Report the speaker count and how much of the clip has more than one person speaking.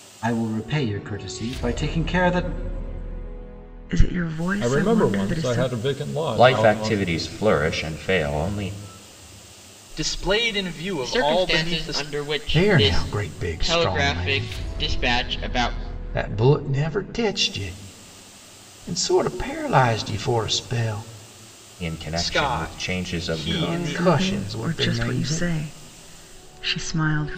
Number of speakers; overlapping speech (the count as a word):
seven, about 29%